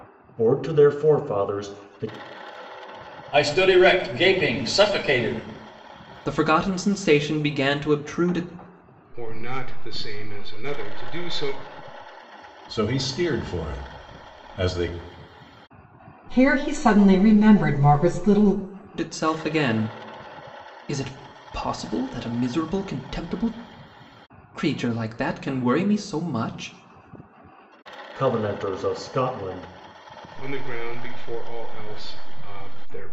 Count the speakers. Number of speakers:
six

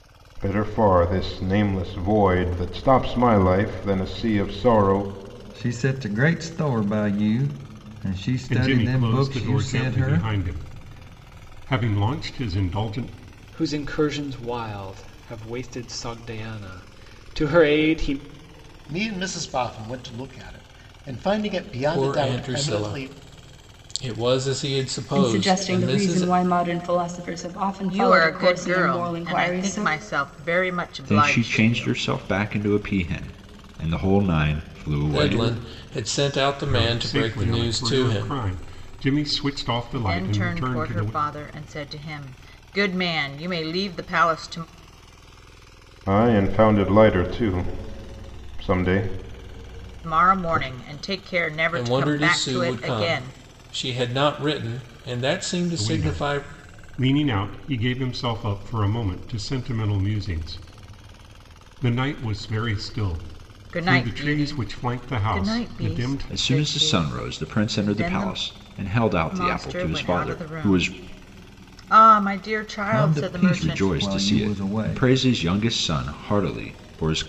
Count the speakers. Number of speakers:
nine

